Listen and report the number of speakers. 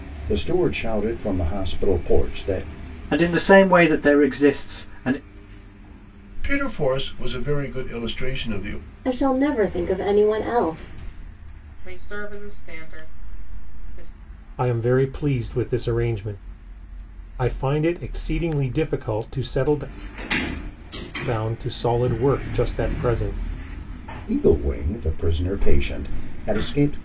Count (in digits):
6